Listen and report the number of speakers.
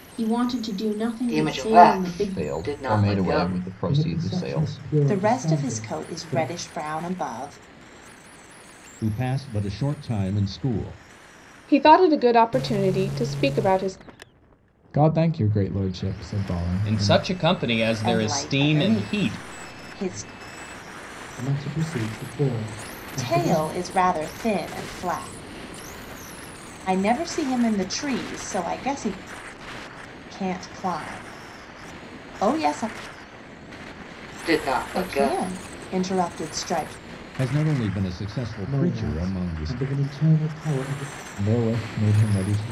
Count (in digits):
9